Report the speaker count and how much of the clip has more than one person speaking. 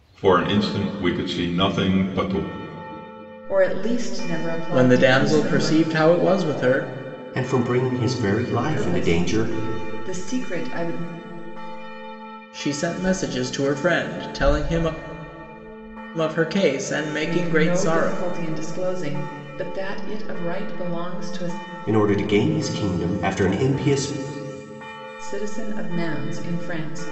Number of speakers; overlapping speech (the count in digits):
4, about 11%